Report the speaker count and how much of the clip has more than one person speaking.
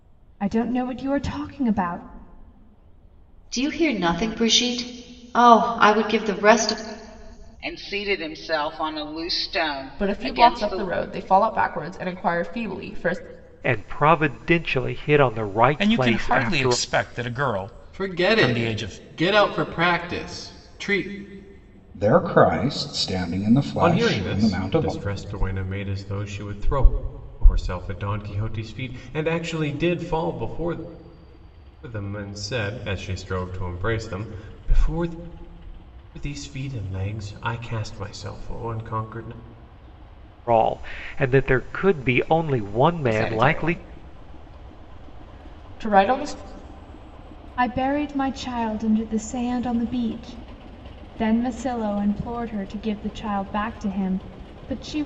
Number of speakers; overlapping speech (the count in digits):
9, about 9%